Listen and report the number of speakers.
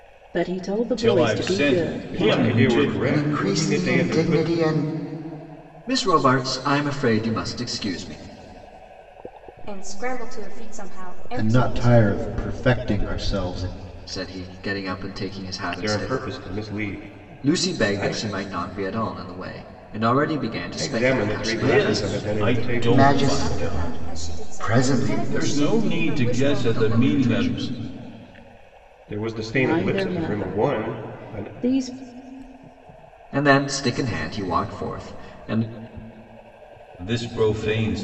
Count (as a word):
seven